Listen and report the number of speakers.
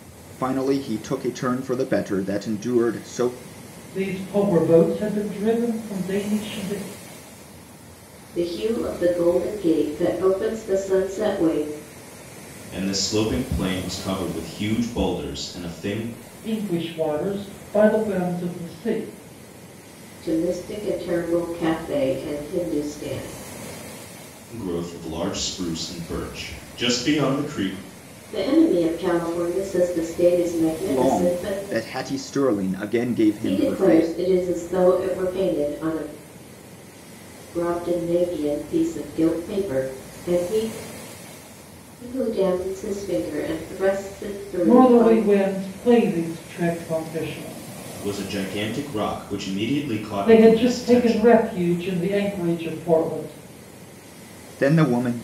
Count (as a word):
four